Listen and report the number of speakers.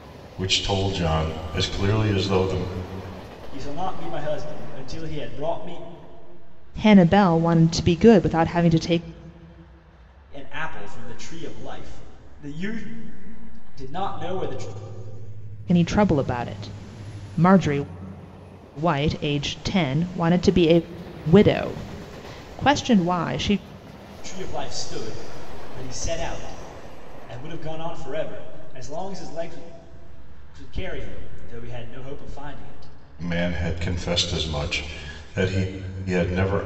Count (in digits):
3